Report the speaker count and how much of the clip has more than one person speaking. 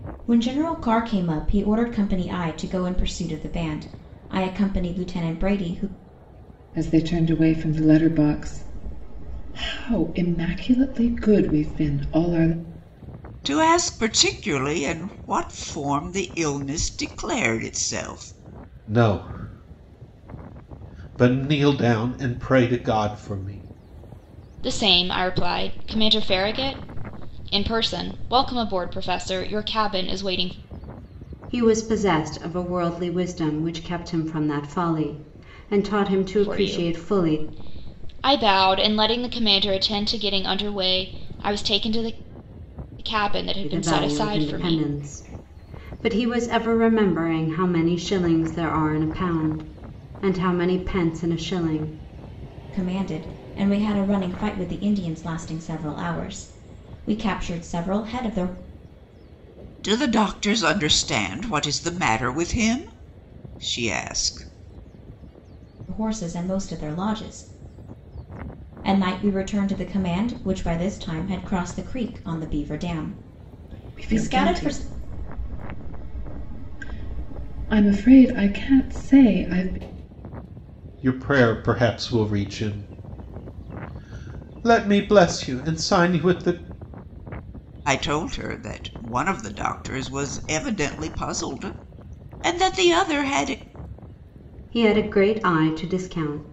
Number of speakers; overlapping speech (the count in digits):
6, about 3%